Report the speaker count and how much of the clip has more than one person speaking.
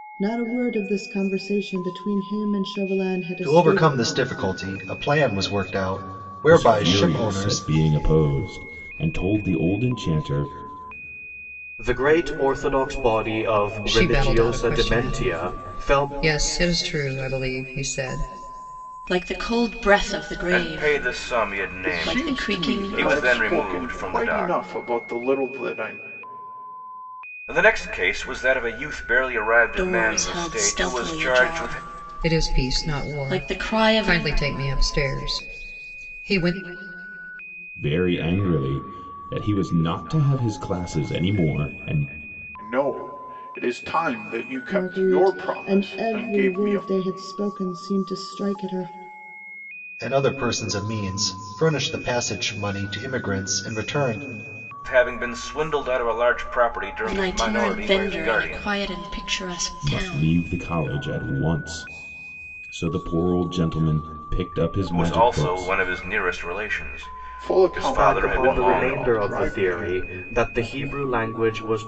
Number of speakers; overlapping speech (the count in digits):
8, about 29%